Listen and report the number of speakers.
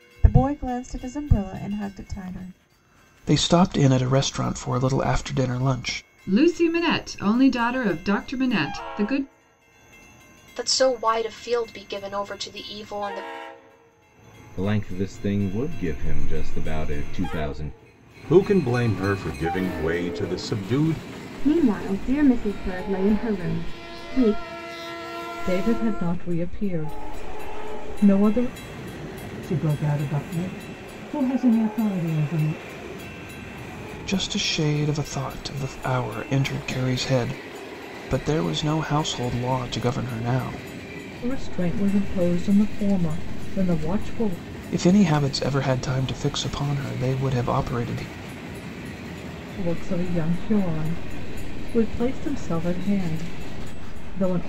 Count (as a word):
nine